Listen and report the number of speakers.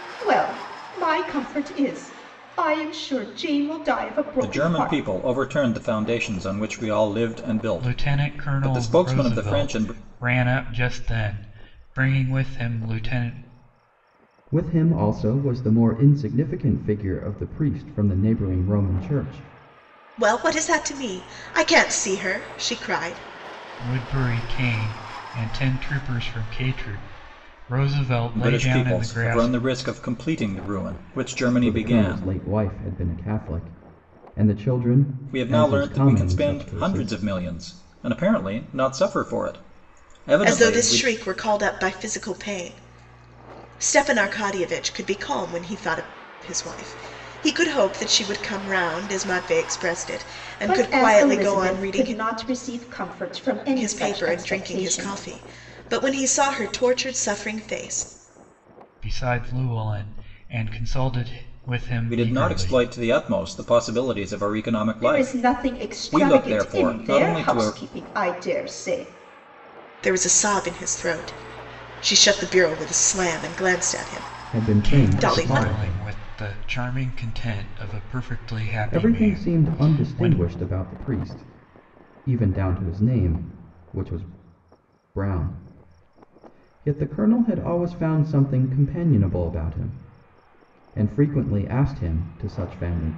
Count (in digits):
5